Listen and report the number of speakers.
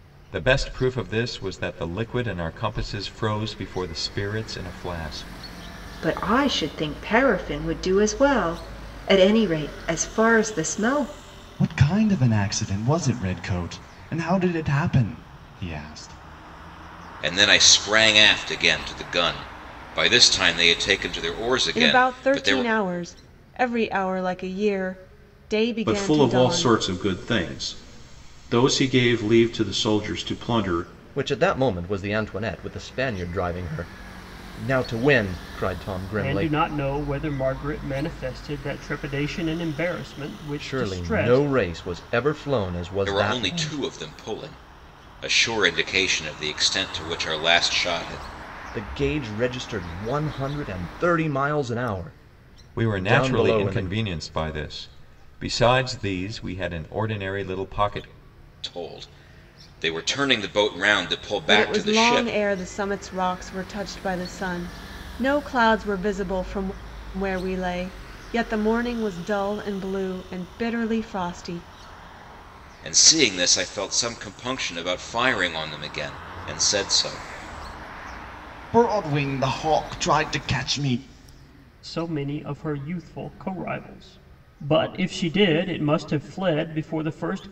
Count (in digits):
8